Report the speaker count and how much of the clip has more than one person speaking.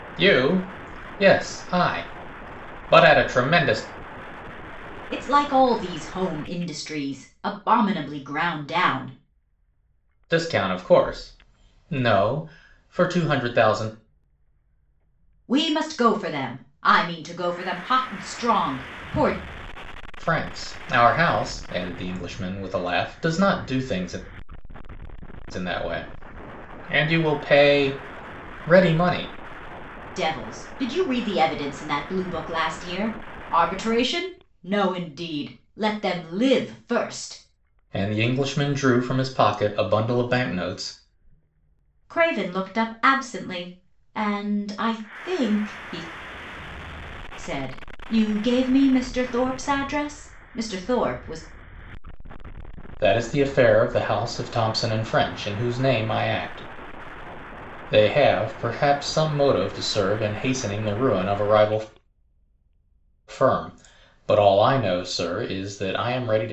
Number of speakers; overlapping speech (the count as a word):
two, no overlap